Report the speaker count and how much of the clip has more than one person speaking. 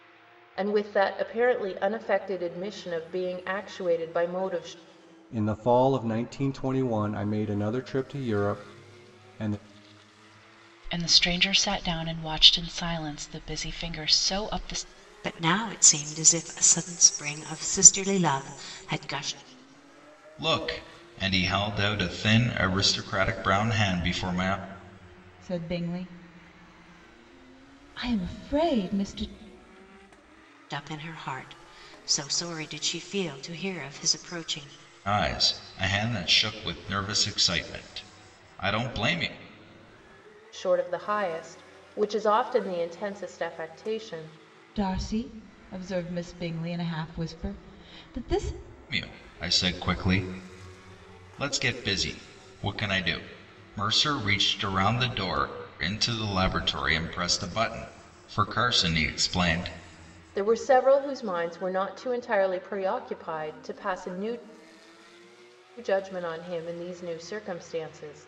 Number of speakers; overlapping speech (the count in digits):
6, no overlap